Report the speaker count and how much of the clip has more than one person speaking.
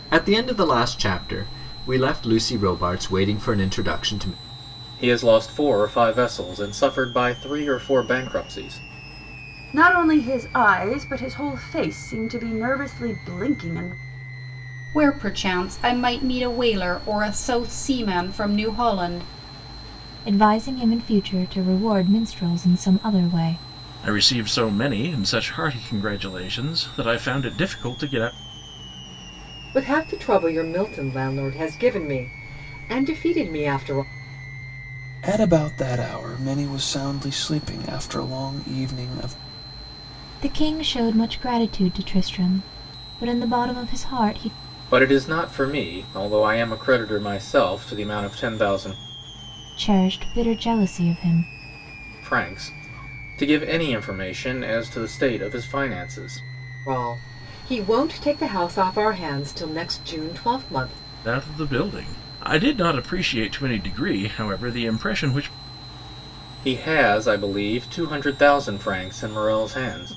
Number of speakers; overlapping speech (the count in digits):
8, no overlap